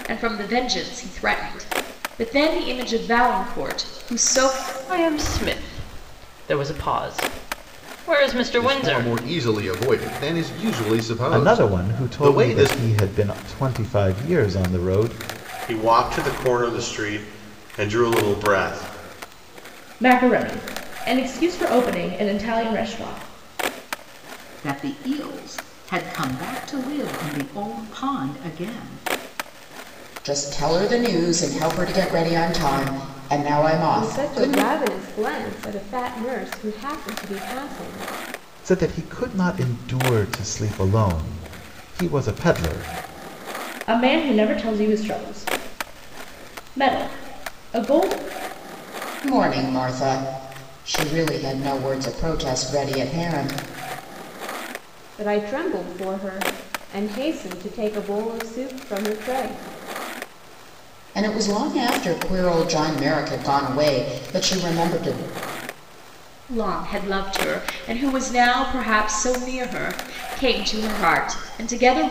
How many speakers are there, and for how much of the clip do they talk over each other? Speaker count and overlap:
9, about 4%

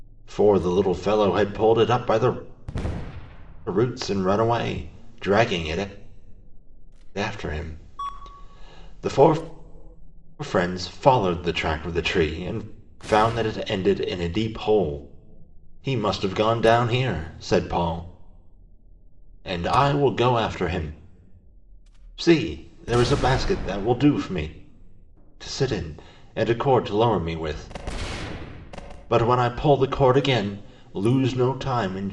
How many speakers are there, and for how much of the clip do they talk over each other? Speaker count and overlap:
1, no overlap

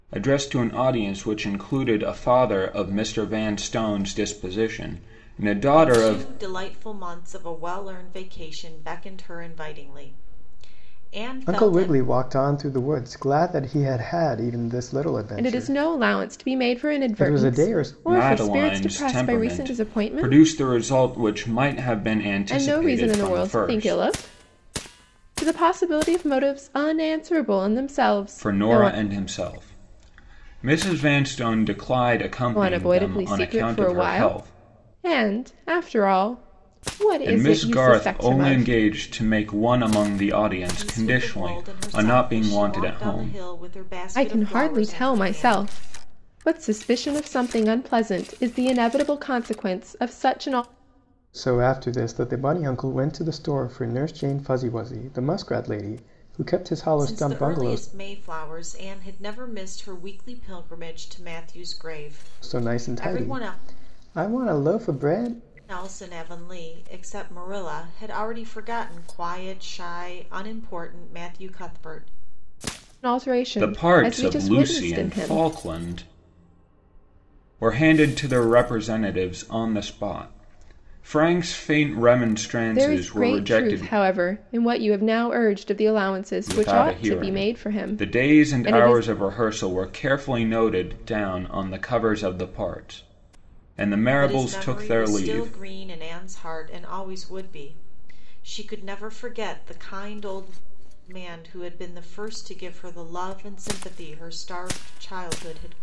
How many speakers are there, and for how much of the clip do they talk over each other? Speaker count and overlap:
4, about 24%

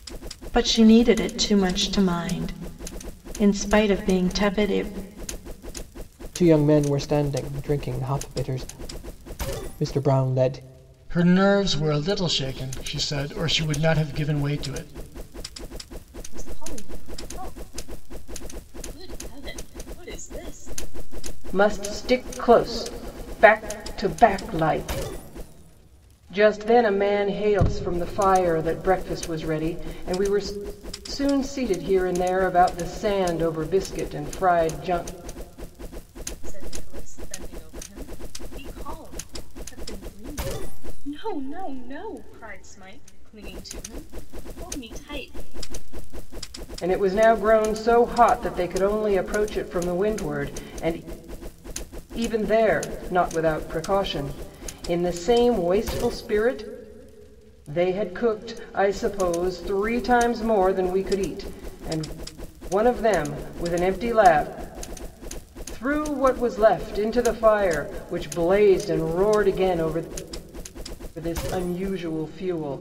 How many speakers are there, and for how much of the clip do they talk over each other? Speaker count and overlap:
5, no overlap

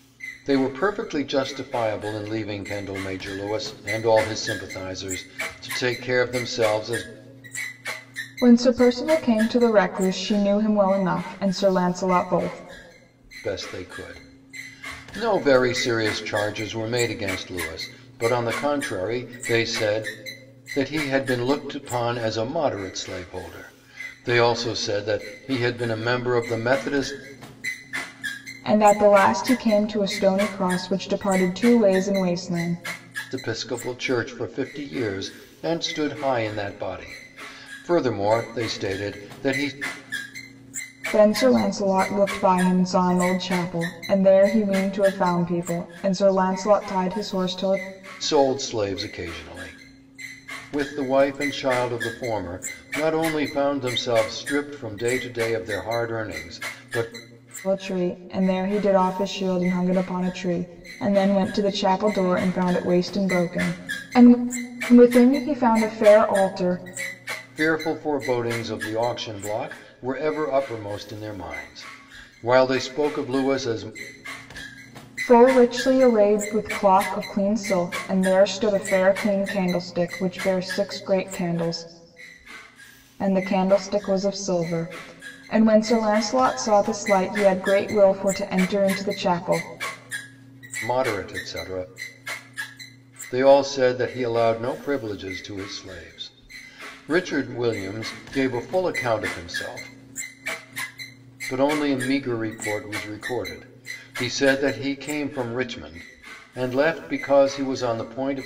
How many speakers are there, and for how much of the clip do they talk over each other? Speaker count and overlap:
2, no overlap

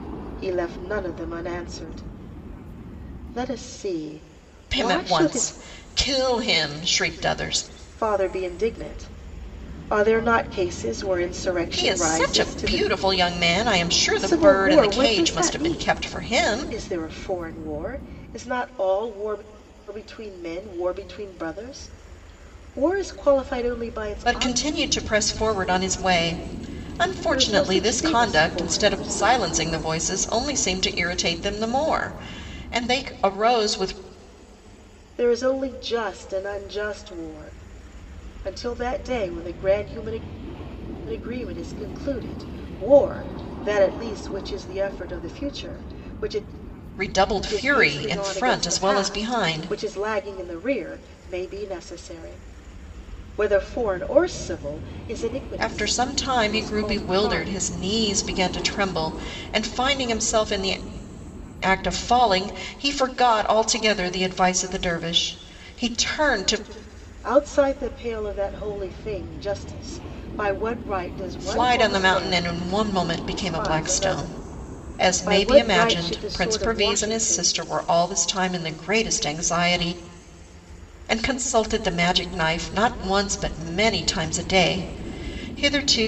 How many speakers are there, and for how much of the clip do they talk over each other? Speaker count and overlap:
2, about 20%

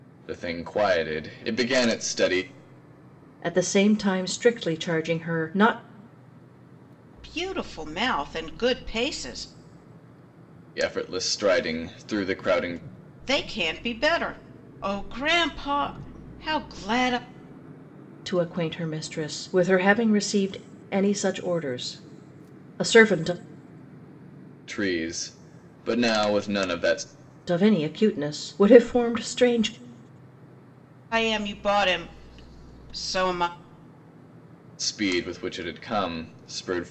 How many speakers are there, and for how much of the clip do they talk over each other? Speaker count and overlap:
3, no overlap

